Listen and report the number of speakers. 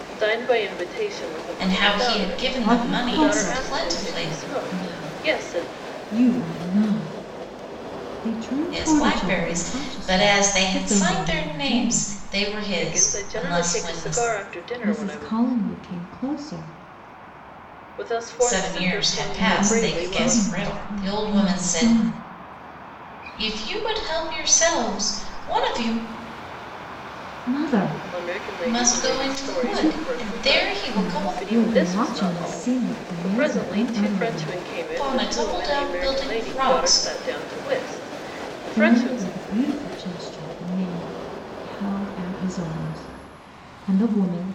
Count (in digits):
3